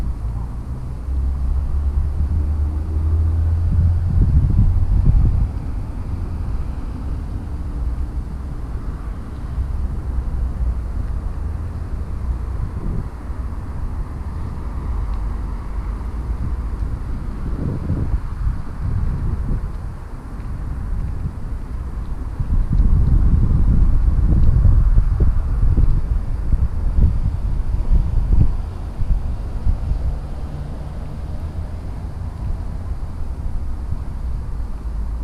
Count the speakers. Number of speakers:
0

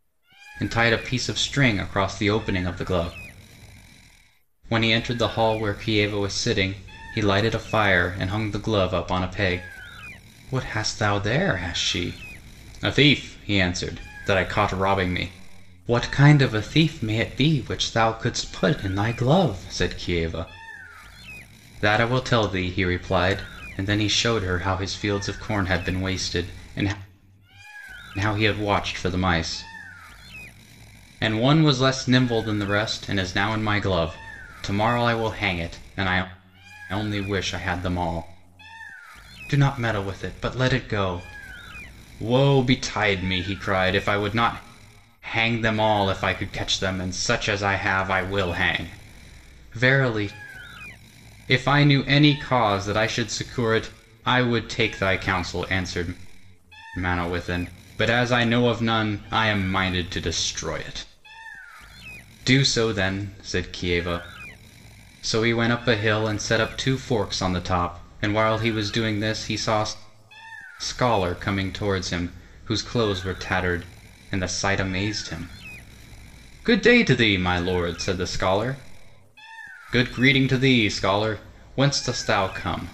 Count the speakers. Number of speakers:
1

